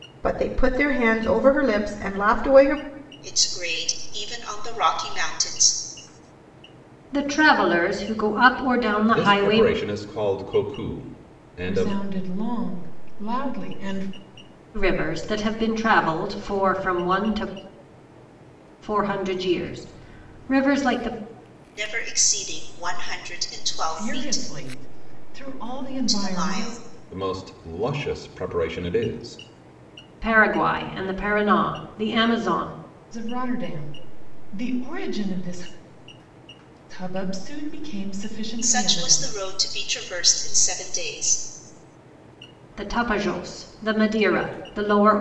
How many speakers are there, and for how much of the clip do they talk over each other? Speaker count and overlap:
5, about 6%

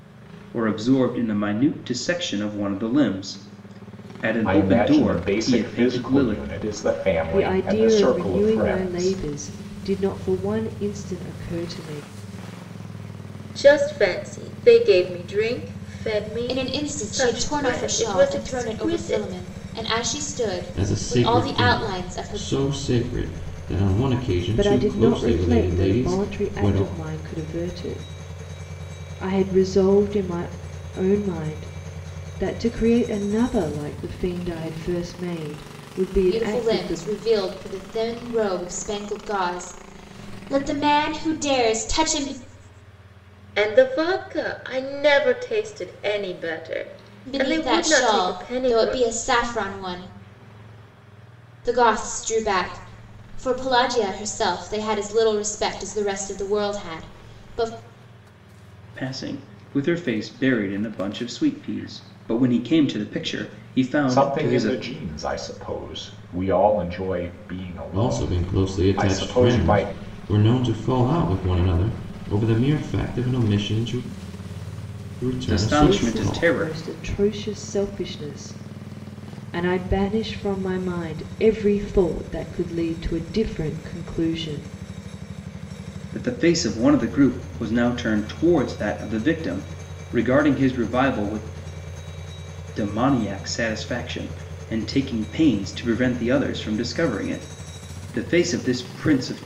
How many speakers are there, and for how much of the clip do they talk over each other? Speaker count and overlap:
6, about 18%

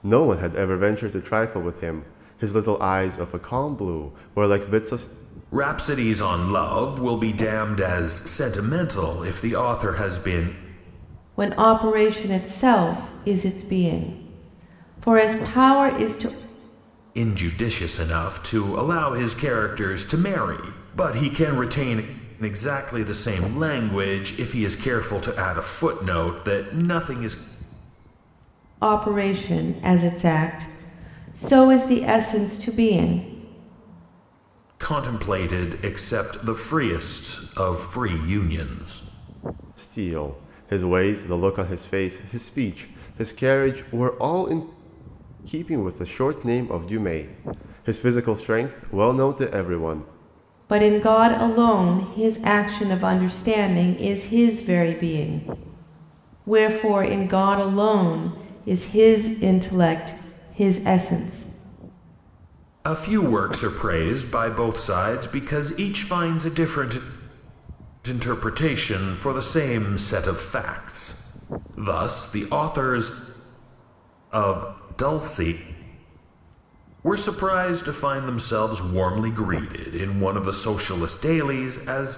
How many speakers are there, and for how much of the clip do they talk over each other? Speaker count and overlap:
3, no overlap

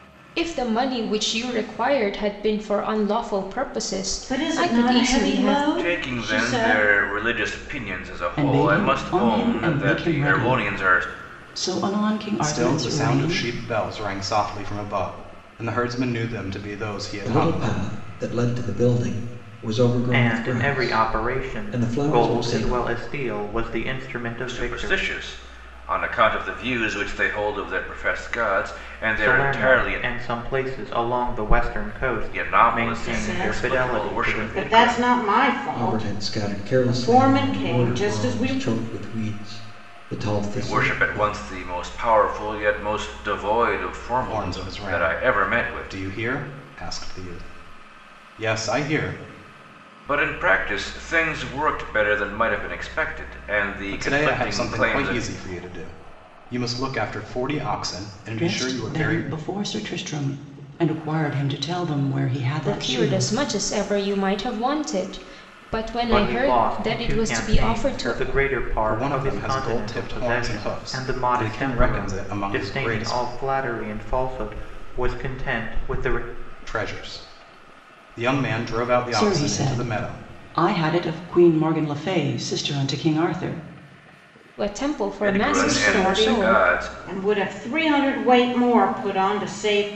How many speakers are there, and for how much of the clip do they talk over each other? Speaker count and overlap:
7, about 36%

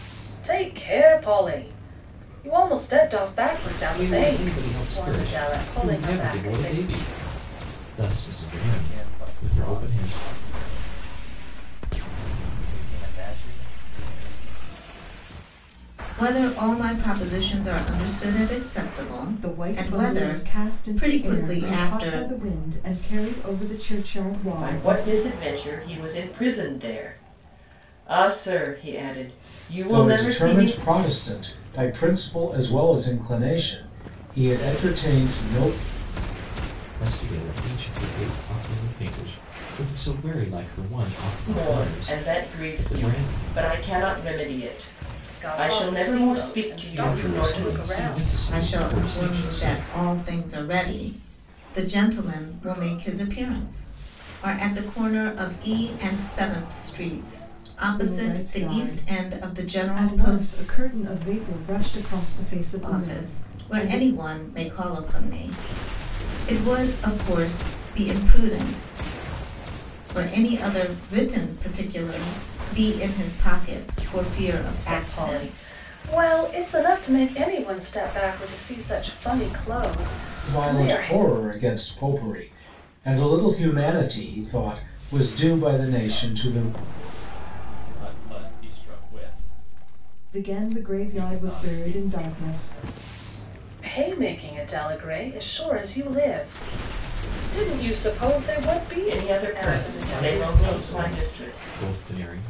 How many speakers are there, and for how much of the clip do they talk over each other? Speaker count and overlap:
7, about 25%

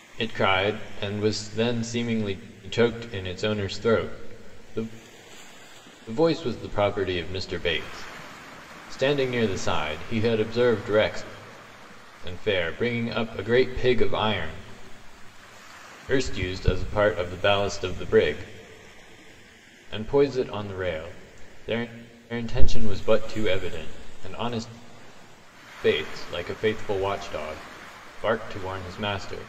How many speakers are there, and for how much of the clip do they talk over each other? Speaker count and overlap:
1, no overlap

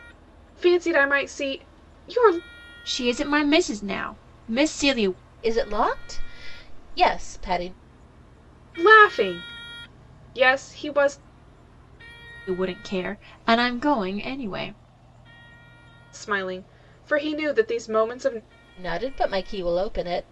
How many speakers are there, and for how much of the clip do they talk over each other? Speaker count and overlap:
3, no overlap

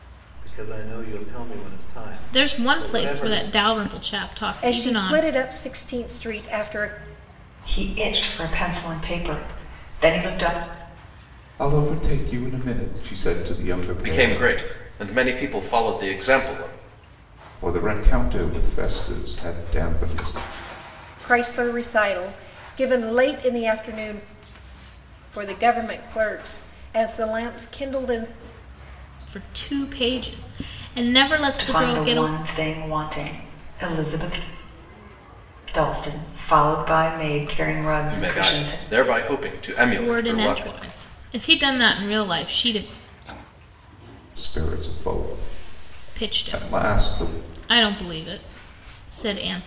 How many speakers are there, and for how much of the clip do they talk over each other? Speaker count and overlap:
6, about 12%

